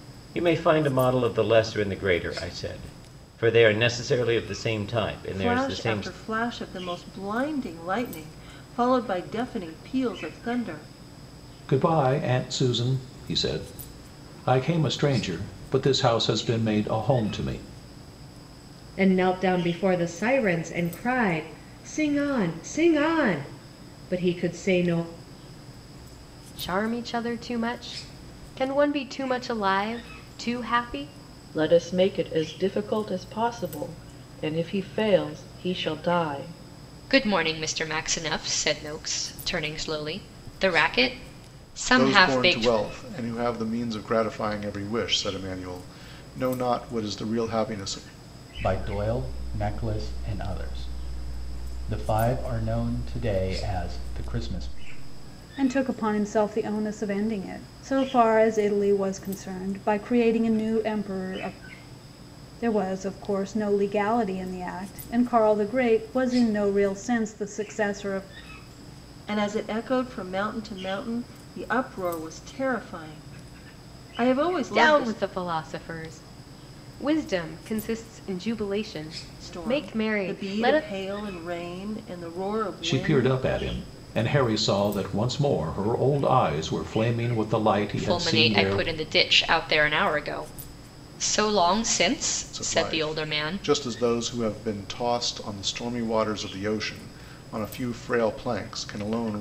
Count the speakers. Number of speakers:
ten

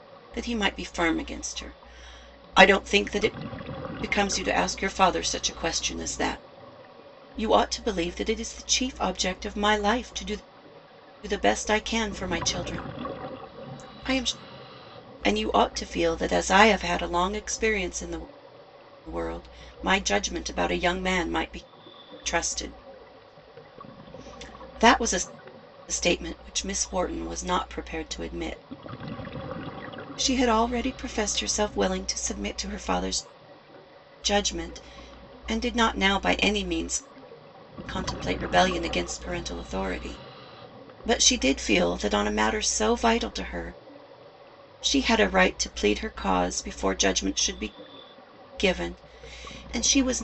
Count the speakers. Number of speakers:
one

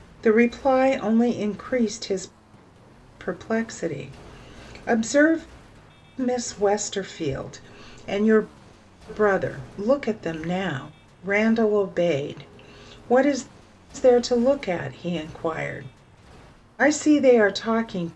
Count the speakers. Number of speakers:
one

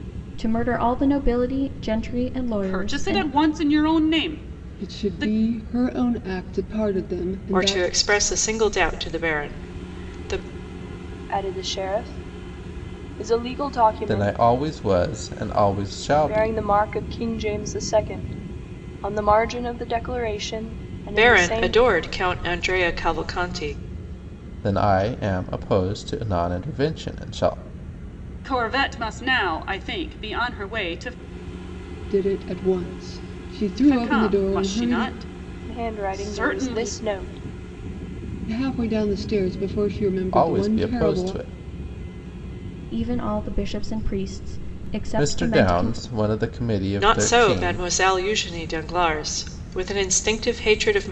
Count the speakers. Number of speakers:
six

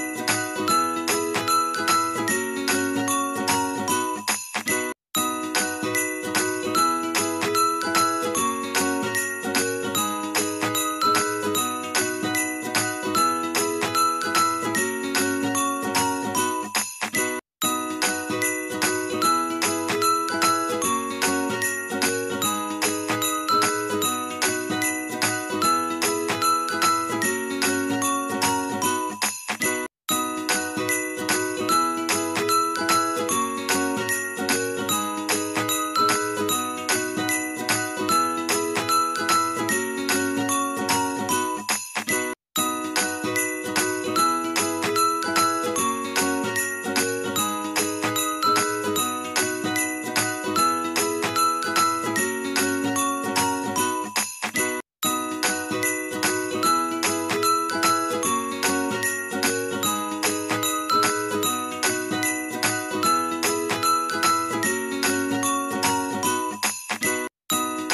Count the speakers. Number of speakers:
zero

